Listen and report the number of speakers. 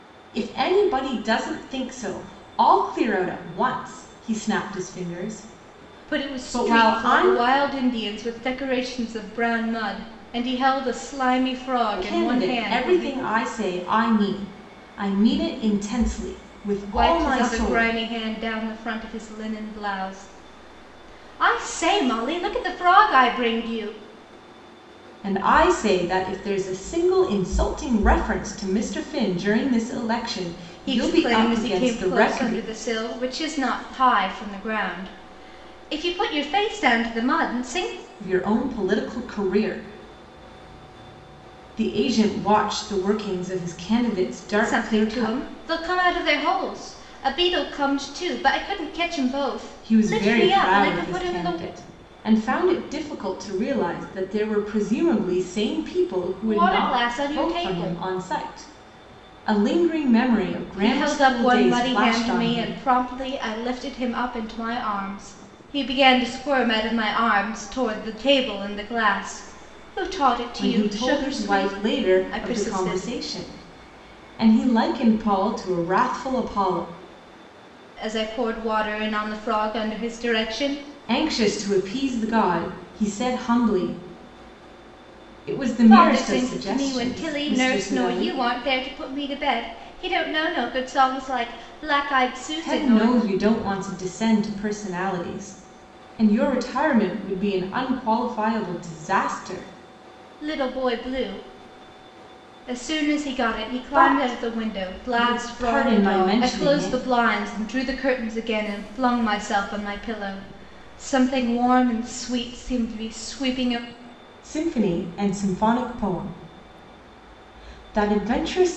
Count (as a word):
two